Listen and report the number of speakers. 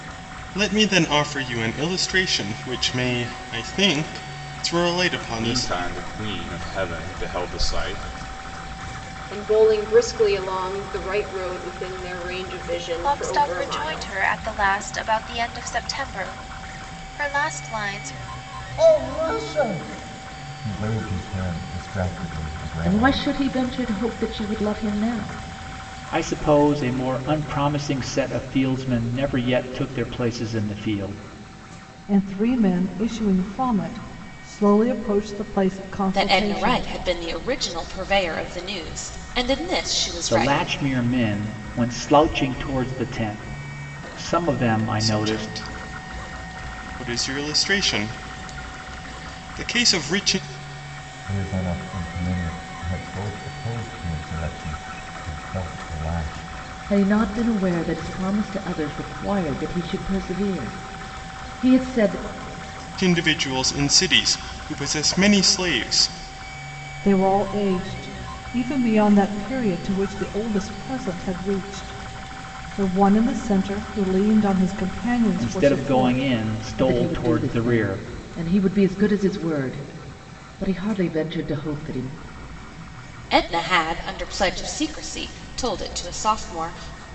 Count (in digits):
9